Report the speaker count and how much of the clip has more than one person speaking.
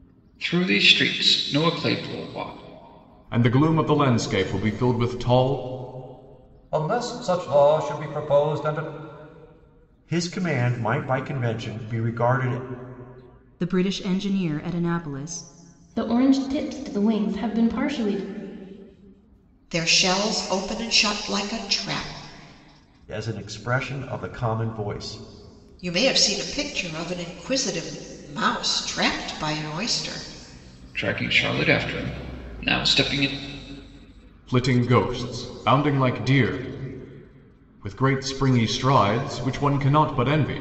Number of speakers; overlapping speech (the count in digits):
7, no overlap